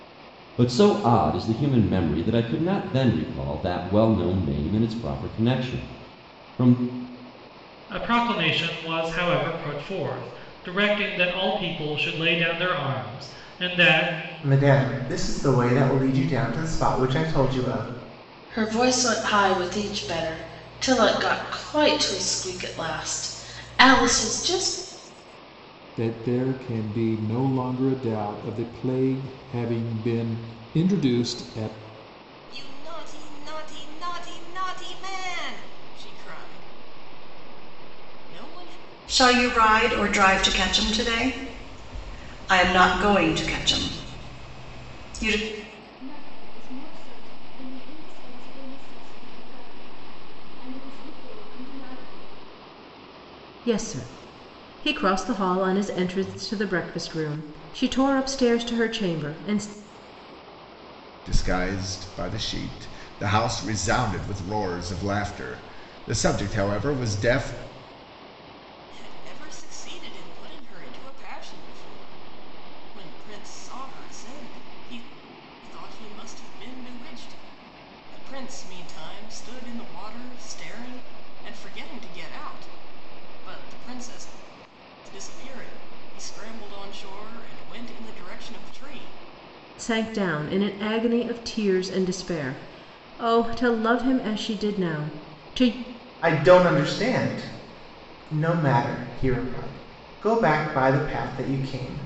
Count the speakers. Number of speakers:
10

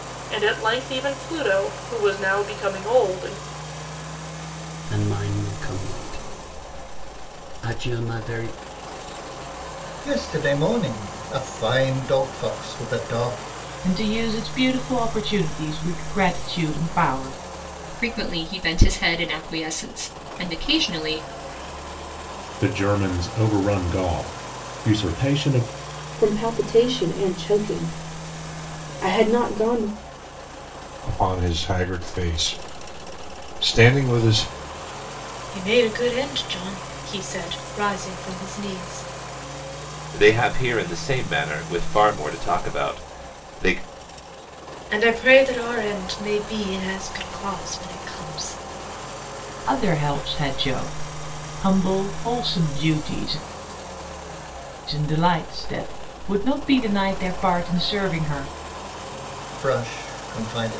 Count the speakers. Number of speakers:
10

